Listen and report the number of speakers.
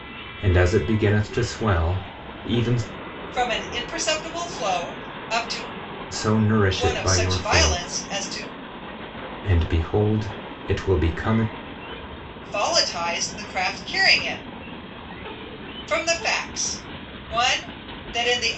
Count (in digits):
2